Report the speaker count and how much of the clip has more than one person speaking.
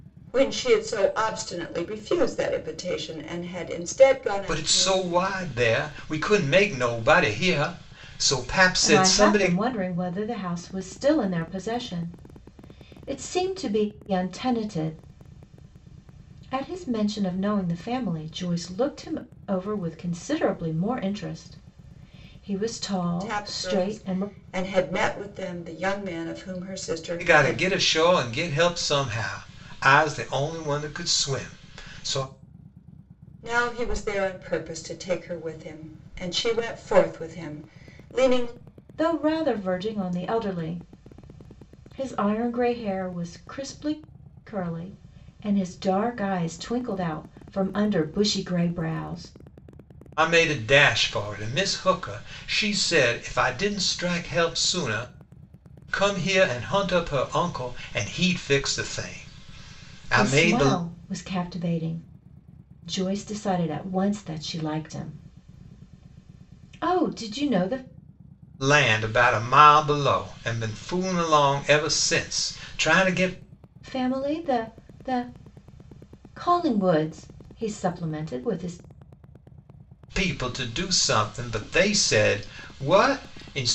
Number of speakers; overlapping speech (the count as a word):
three, about 4%